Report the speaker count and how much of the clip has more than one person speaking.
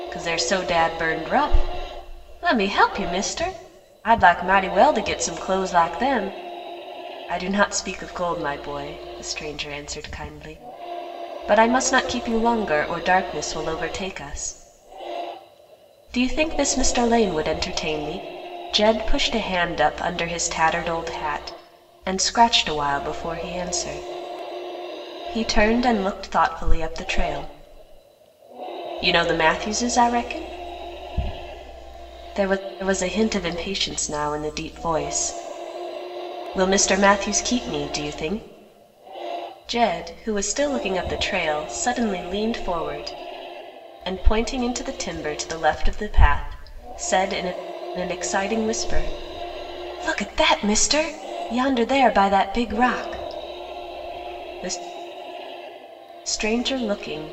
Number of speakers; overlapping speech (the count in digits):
1, no overlap